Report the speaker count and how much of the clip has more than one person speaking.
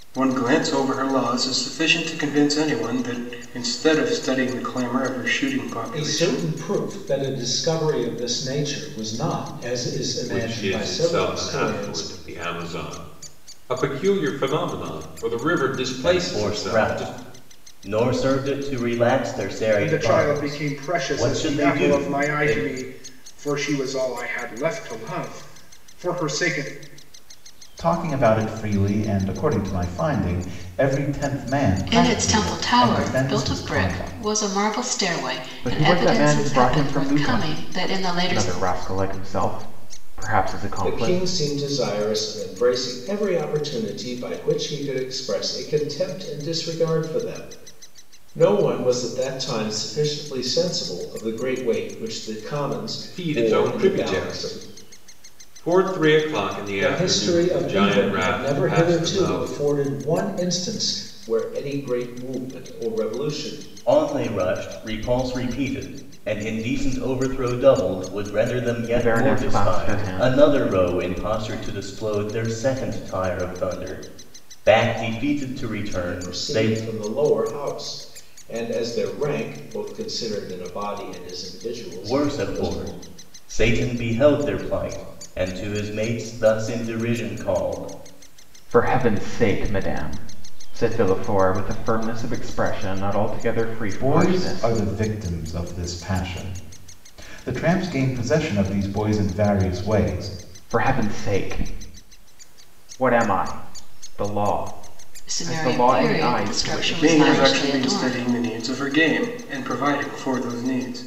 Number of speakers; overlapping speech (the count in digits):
8, about 22%